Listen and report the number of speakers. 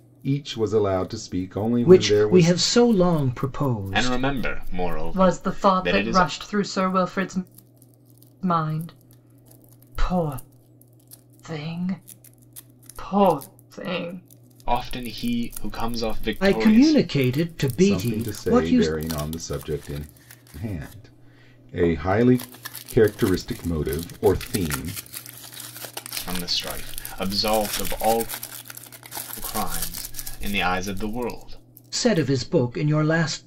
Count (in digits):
4